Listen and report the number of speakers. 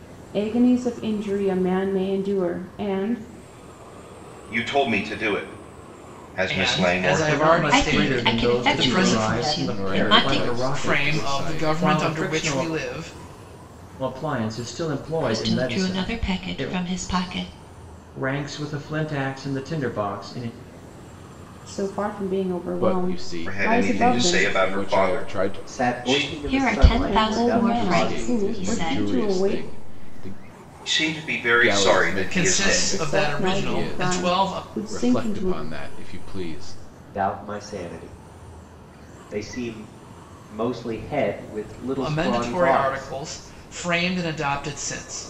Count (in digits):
7